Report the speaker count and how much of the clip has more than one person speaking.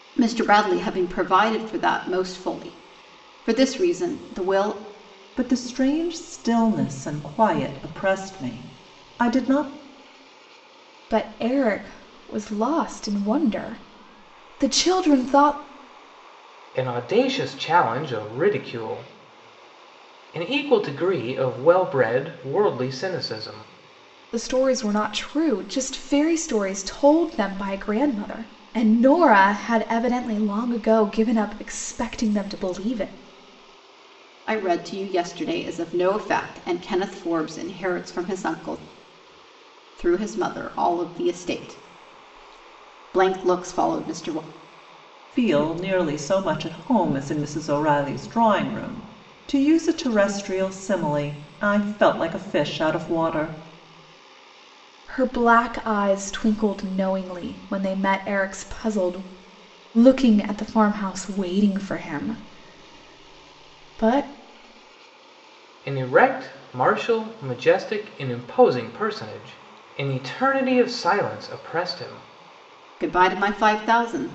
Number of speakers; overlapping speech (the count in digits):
4, no overlap